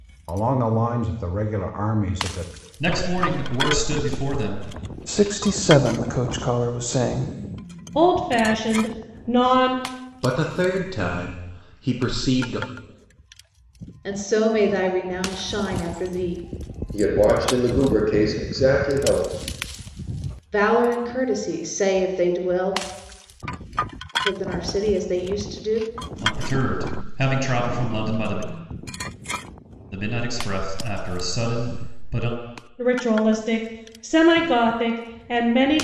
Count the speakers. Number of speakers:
7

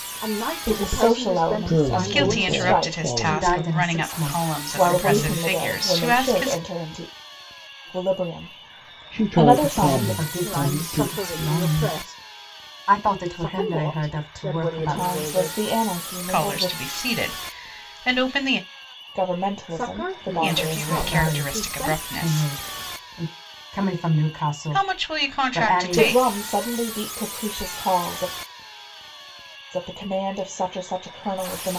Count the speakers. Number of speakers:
5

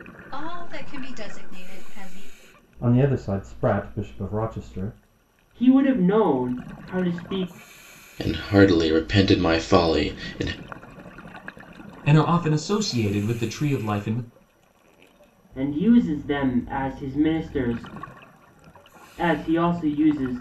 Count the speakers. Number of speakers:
5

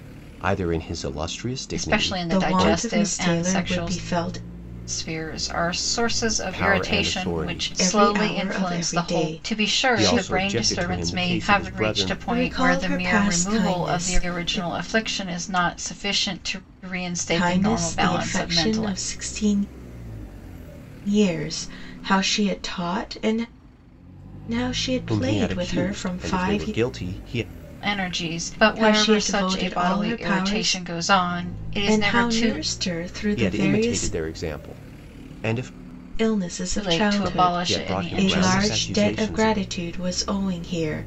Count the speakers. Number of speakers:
3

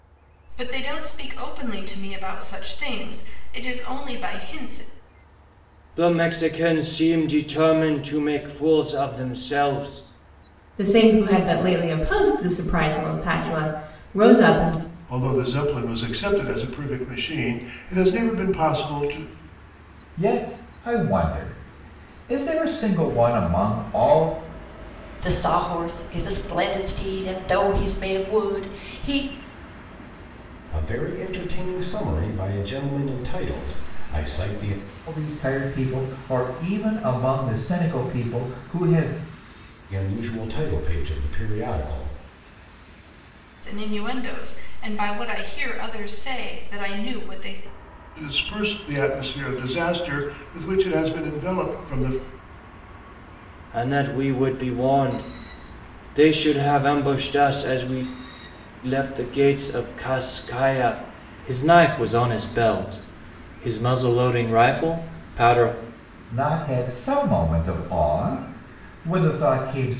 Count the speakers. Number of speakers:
7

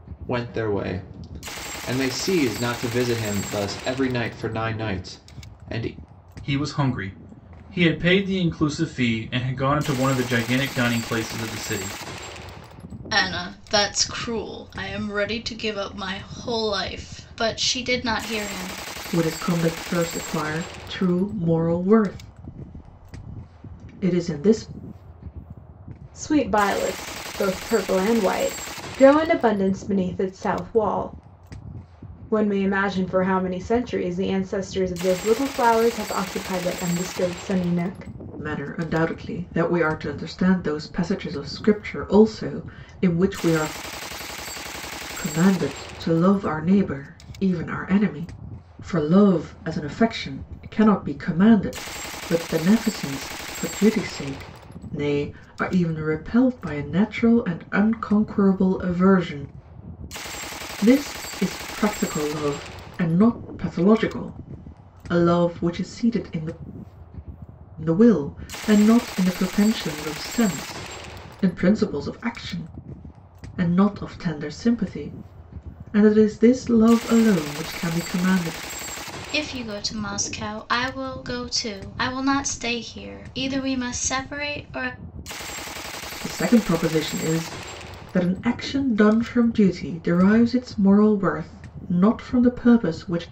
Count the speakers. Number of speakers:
5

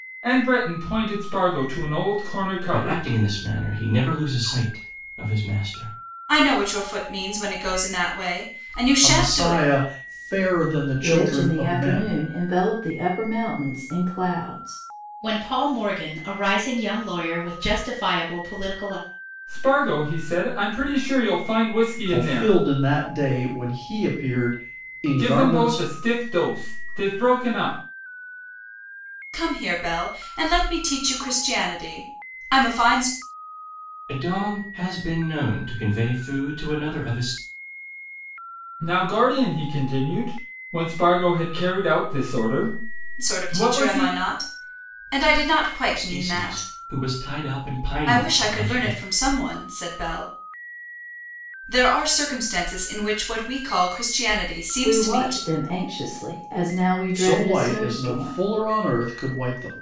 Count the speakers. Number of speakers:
6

